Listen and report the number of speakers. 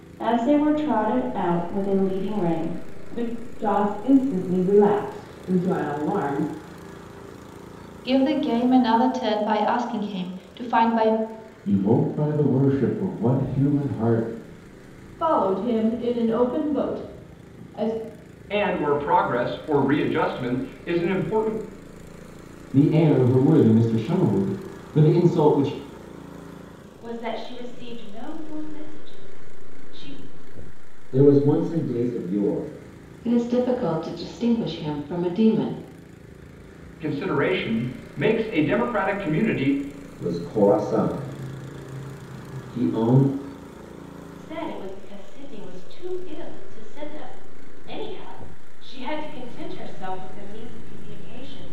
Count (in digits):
10